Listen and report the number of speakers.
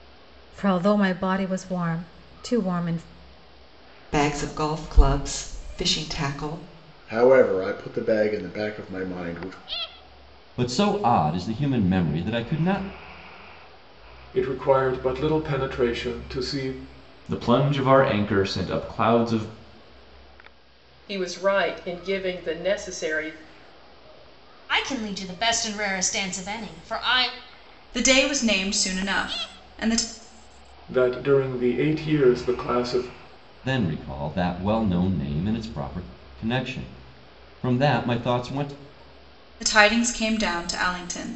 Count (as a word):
nine